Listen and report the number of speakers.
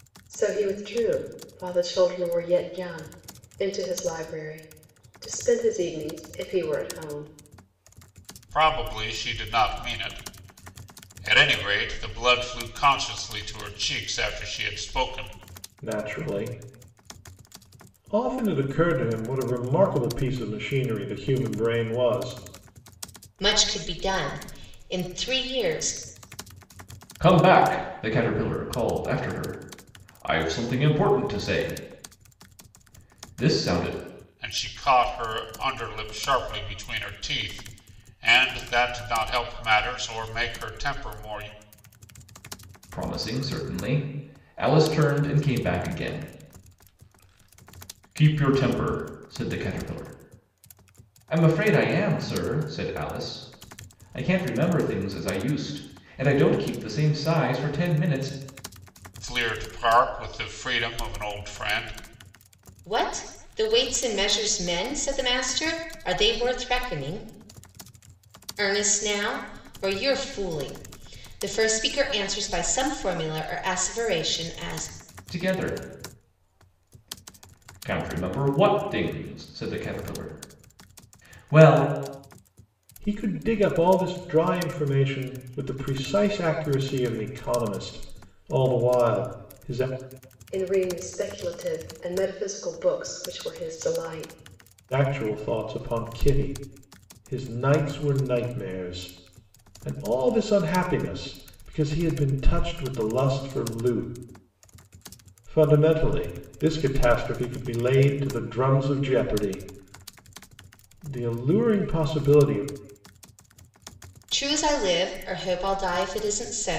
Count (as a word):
five